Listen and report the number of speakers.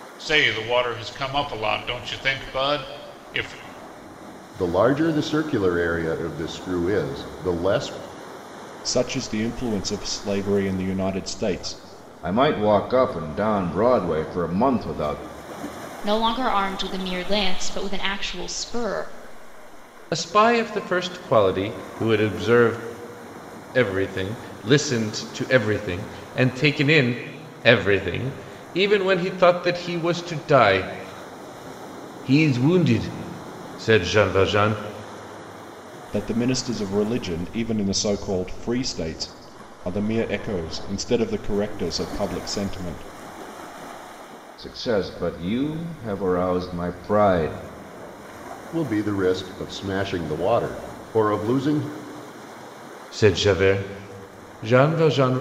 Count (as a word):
six